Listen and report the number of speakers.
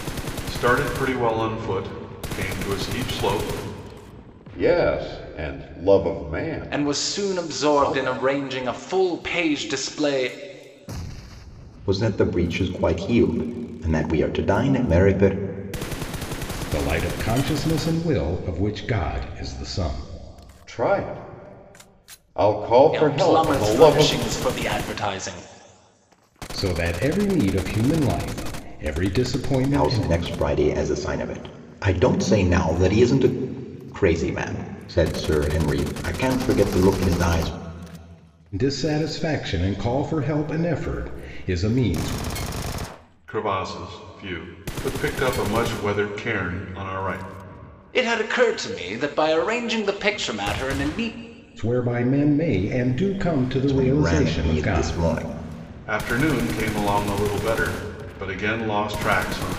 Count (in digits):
5